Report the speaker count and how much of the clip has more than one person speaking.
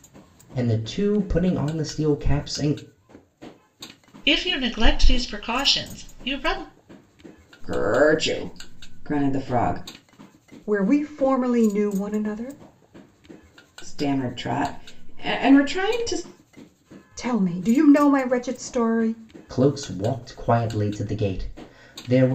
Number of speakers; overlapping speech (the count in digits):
4, no overlap